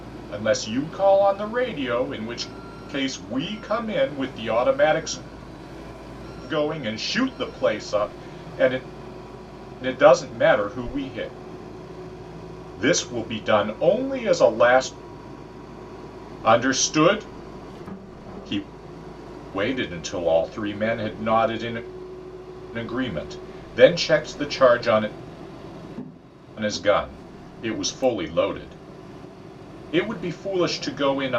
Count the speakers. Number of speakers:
one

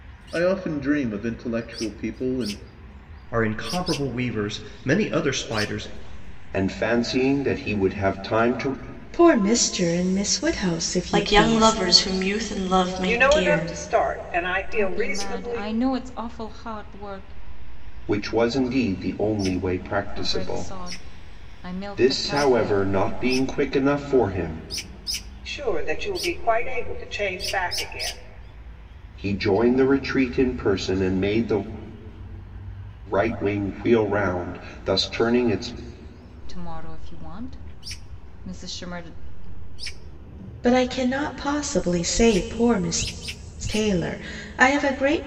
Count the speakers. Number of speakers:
seven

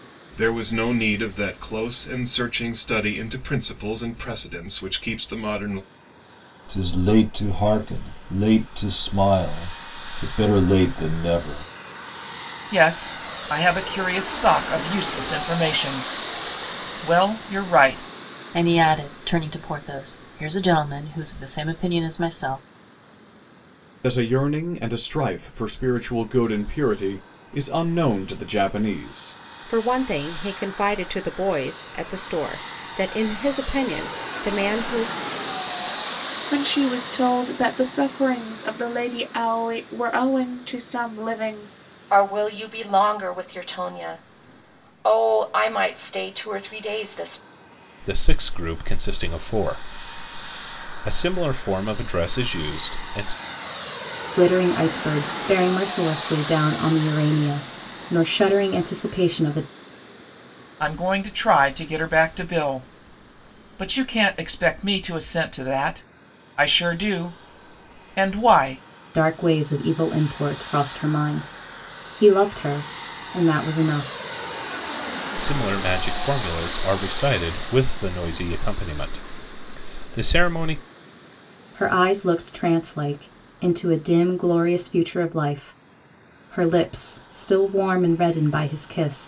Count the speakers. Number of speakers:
ten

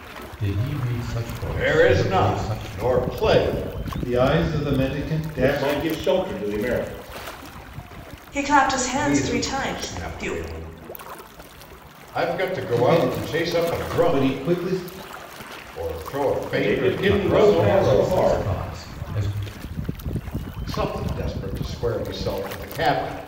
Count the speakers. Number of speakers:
five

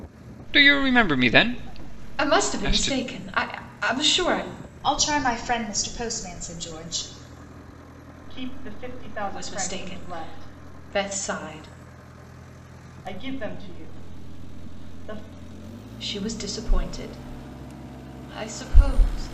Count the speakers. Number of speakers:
four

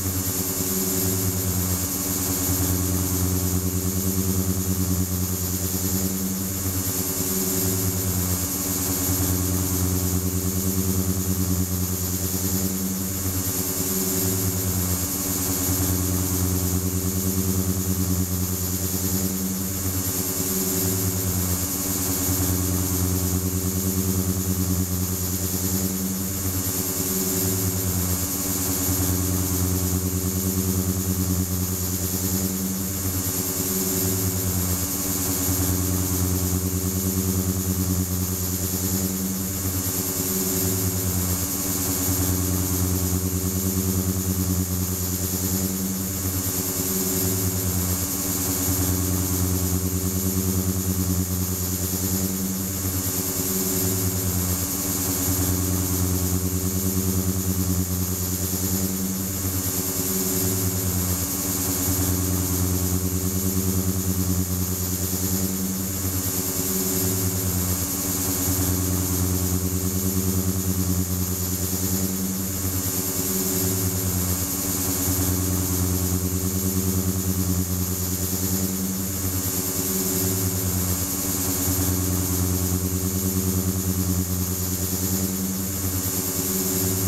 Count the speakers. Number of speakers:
zero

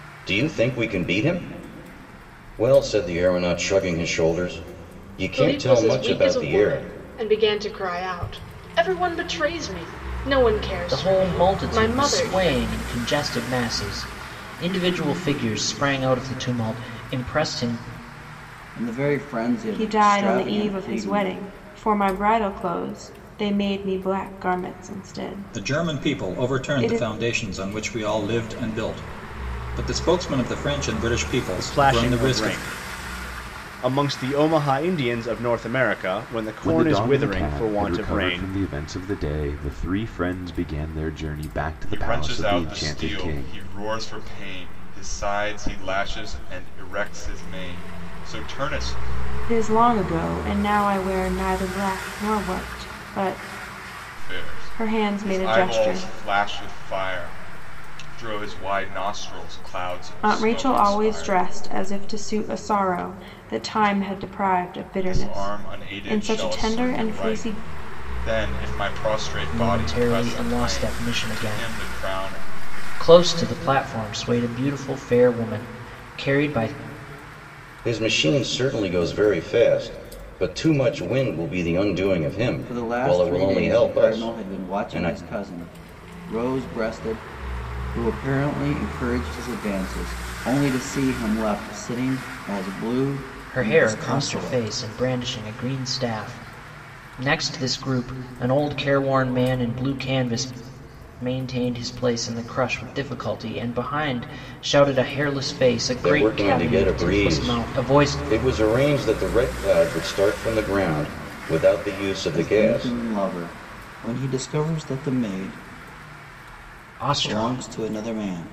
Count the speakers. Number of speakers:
nine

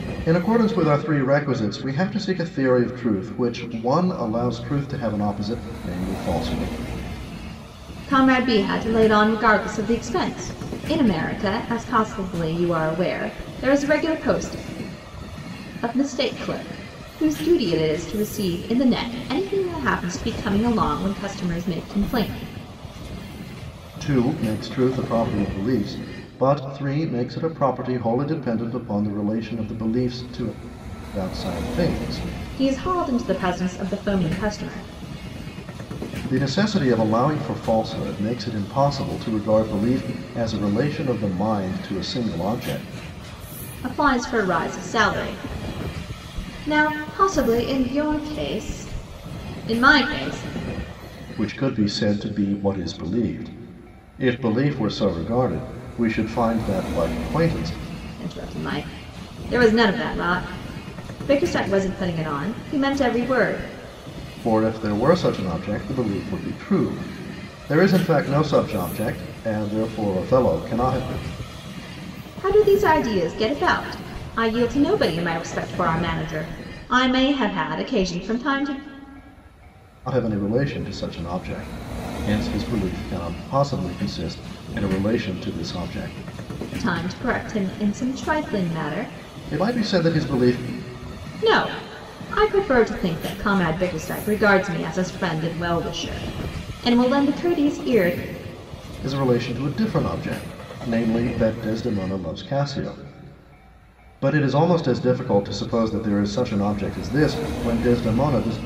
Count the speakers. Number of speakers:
two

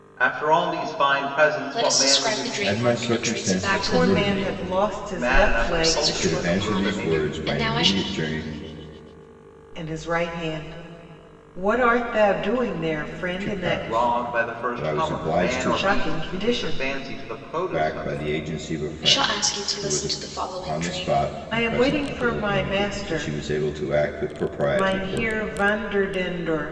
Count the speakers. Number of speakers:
four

